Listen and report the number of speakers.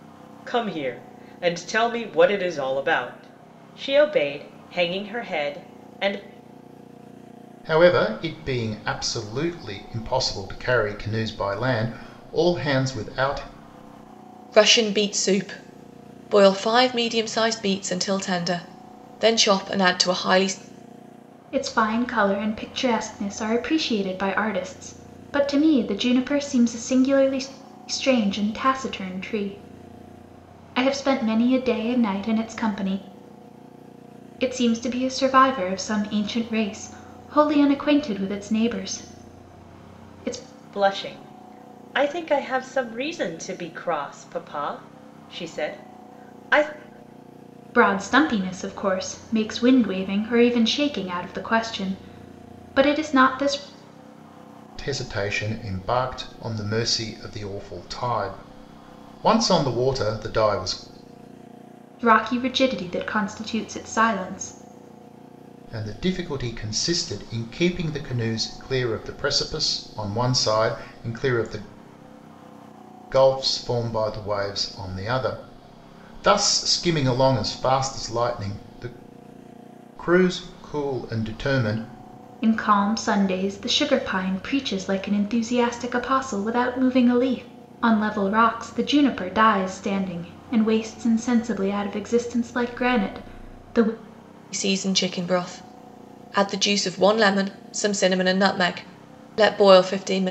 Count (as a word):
four